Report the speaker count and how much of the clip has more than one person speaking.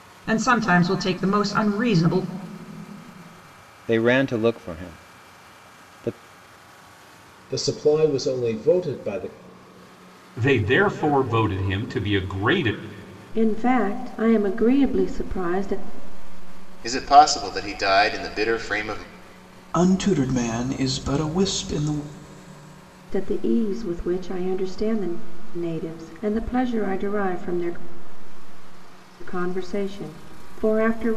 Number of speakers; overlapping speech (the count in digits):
7, no overlap